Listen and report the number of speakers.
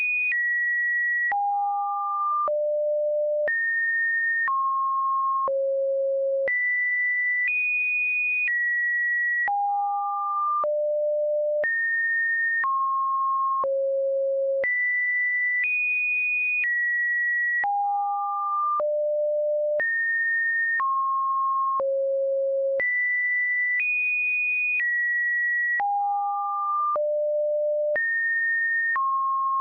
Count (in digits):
0